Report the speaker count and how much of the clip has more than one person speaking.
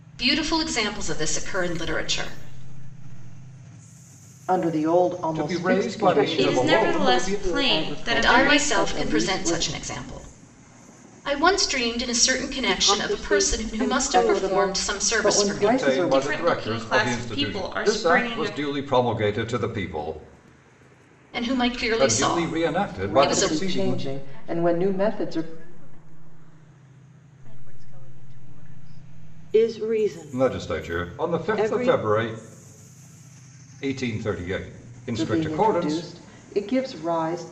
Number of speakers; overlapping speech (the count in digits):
6, about 48%